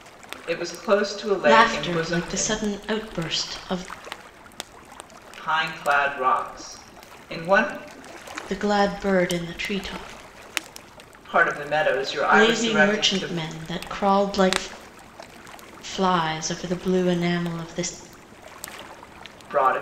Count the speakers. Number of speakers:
2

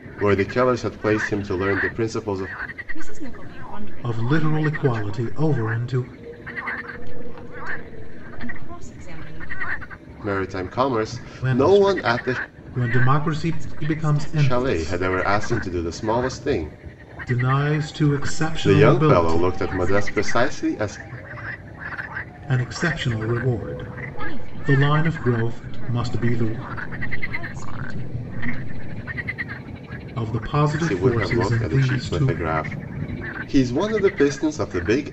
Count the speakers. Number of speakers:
3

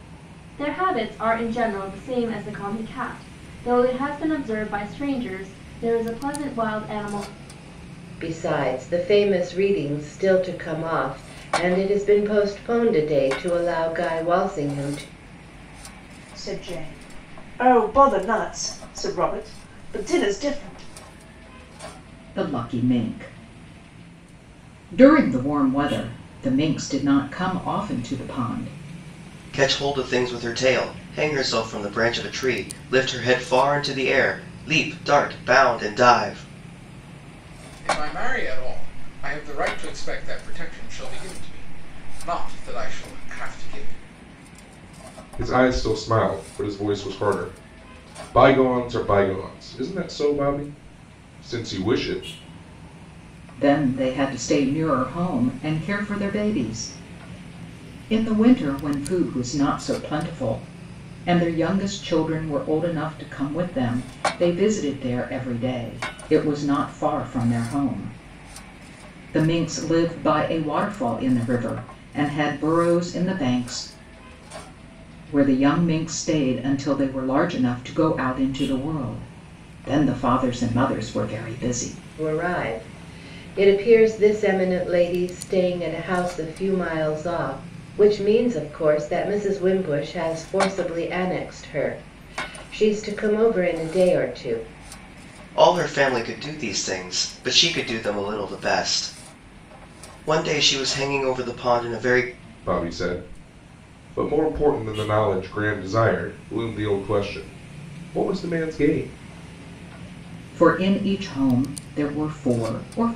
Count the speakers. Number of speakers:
7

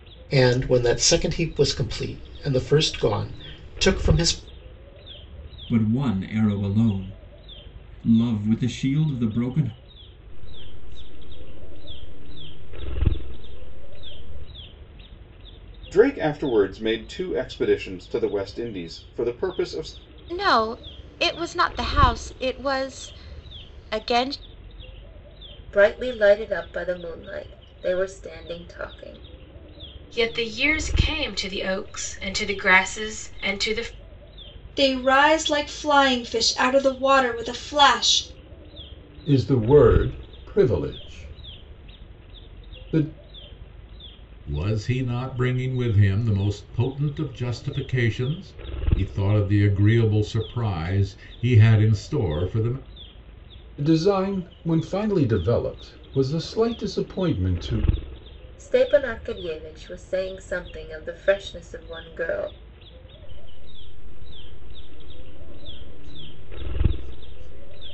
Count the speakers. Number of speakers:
10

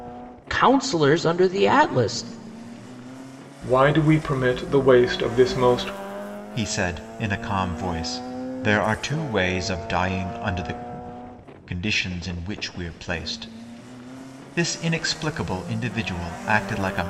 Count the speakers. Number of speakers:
3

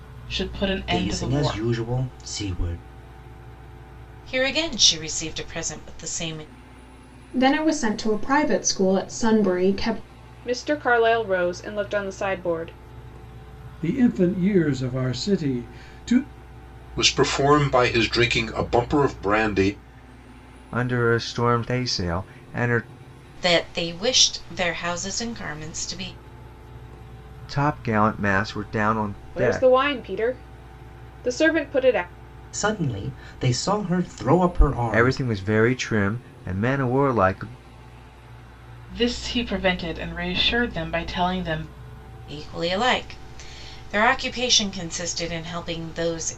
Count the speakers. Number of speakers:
8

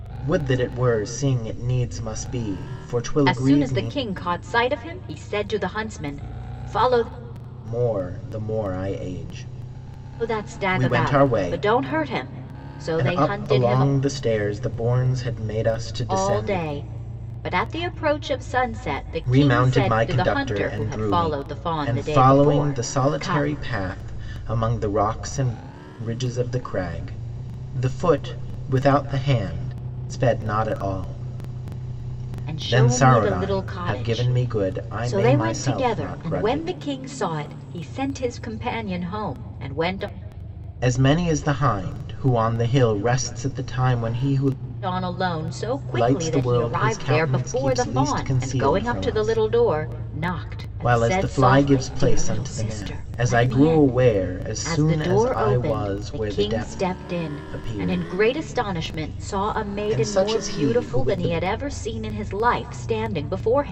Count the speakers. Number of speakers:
2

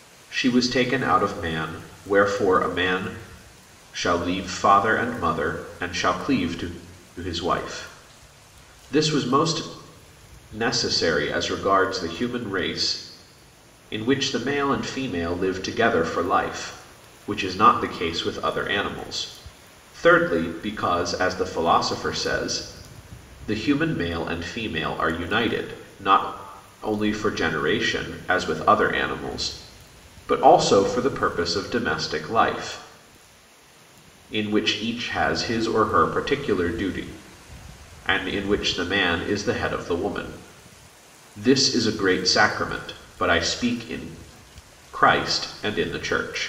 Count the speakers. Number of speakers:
1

